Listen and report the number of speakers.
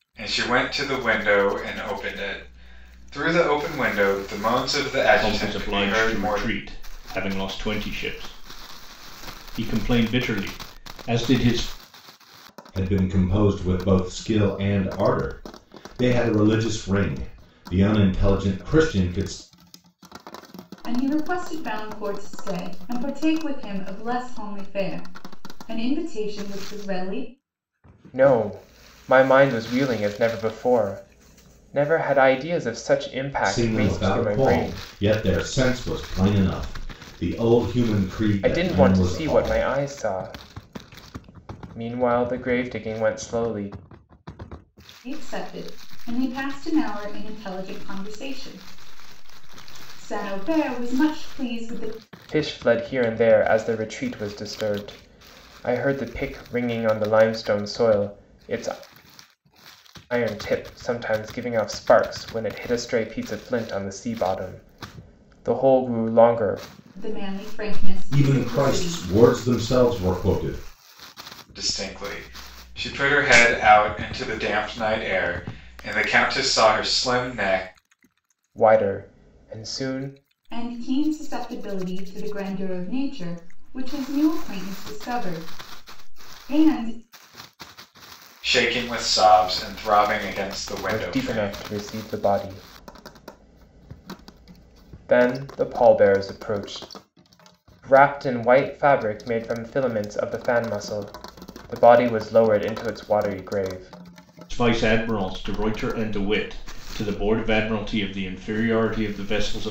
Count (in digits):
5